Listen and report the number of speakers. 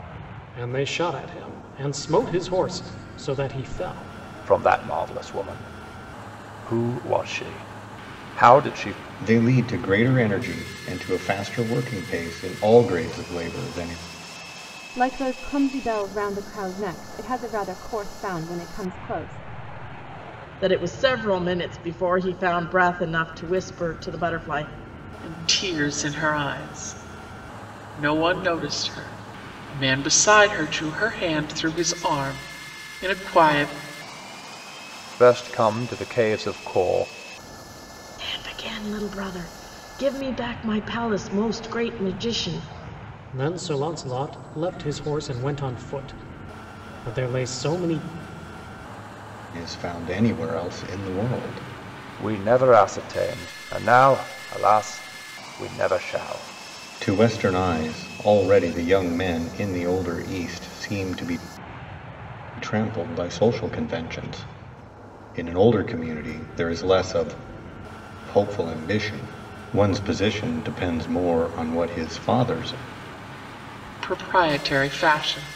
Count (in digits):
6